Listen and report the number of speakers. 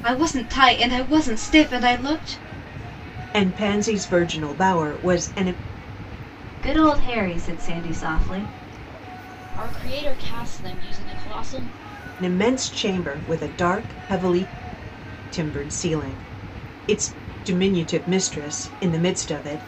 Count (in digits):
4